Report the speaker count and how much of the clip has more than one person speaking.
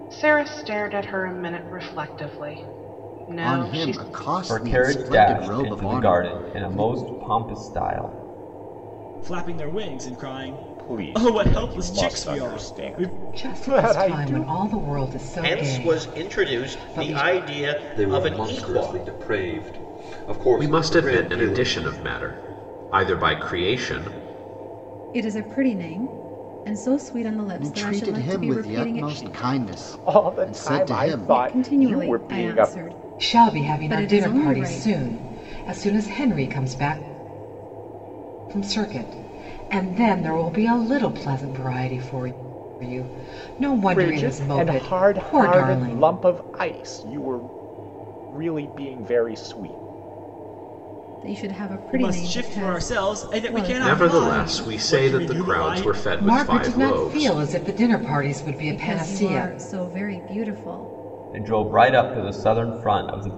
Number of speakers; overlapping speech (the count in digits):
10, about 41%